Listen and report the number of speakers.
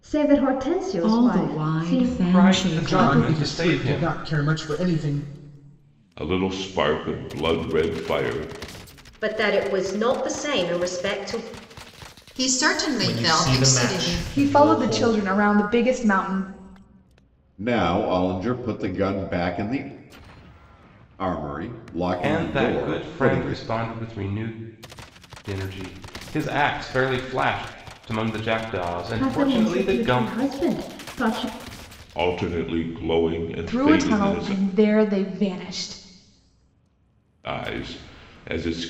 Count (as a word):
ten